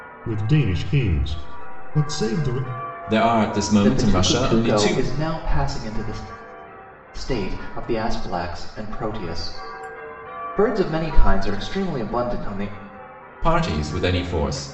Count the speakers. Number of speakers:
three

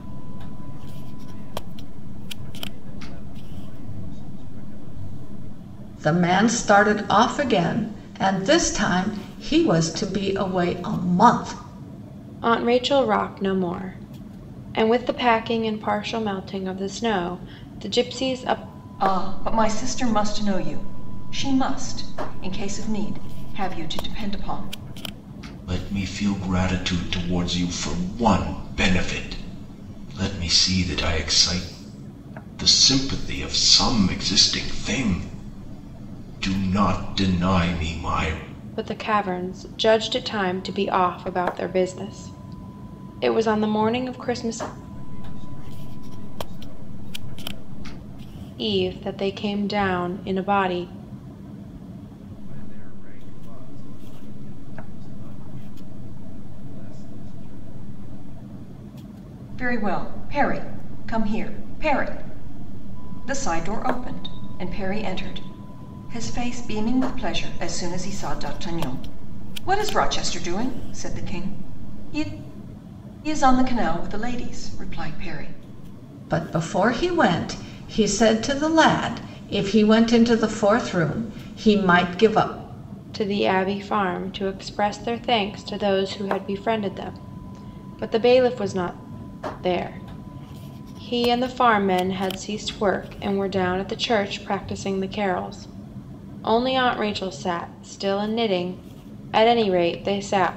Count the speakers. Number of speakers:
five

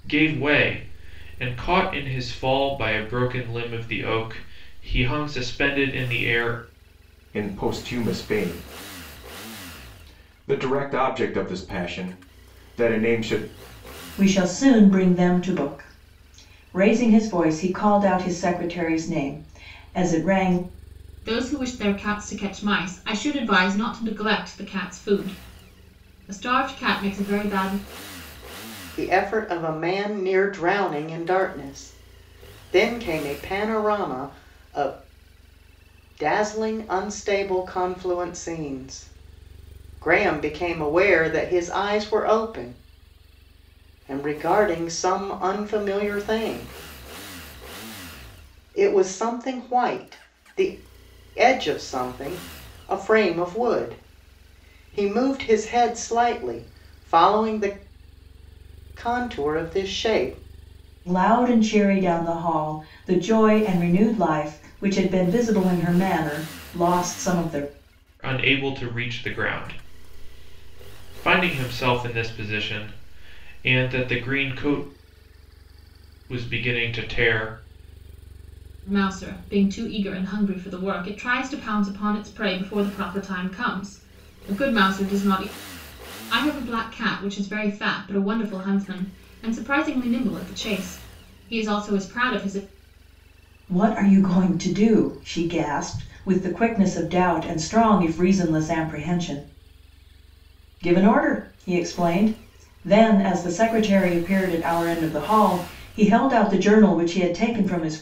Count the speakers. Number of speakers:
five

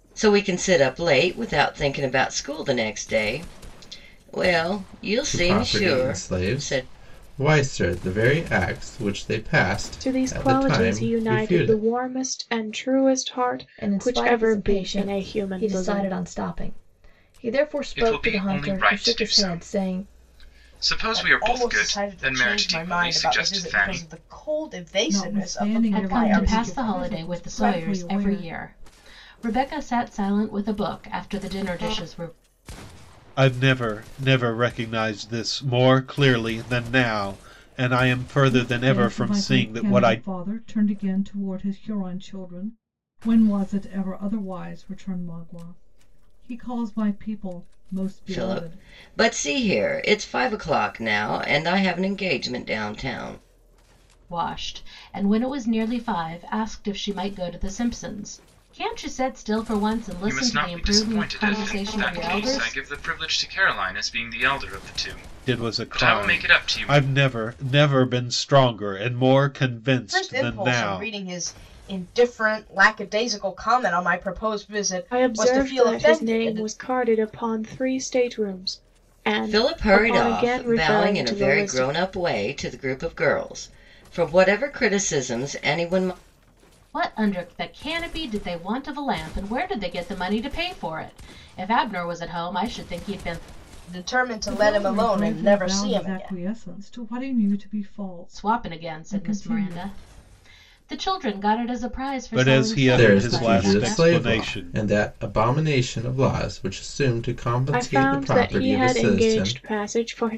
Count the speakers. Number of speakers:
nine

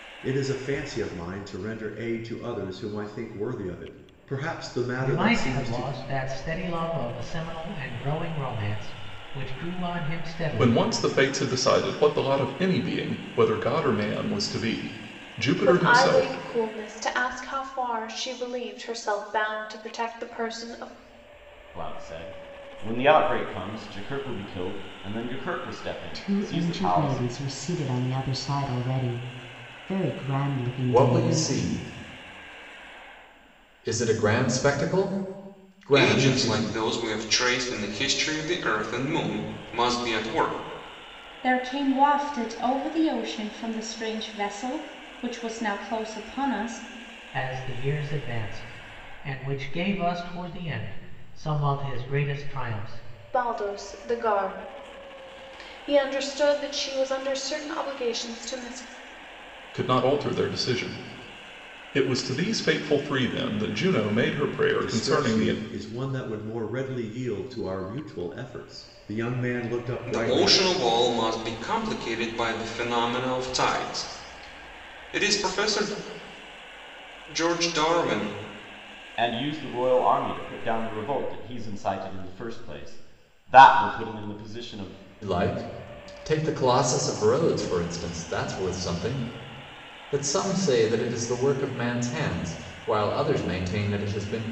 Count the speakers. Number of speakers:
nine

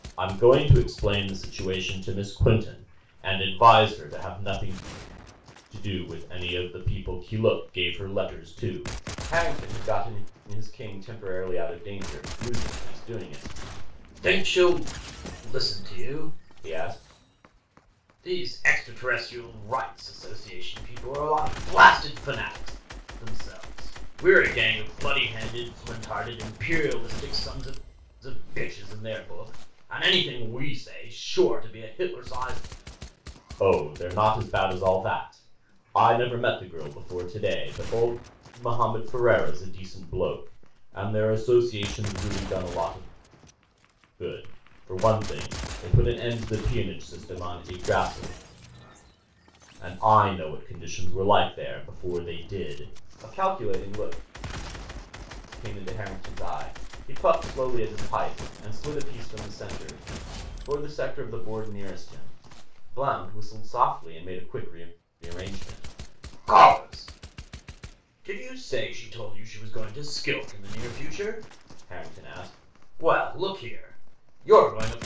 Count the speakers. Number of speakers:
one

